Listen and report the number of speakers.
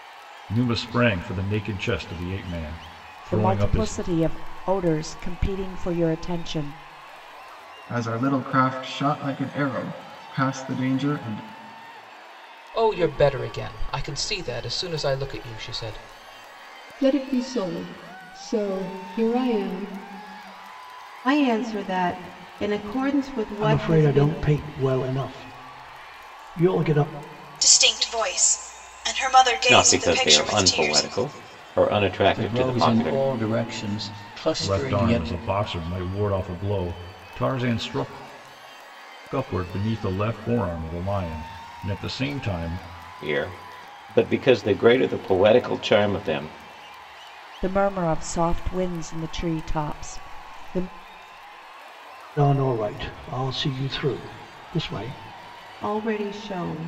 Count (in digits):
10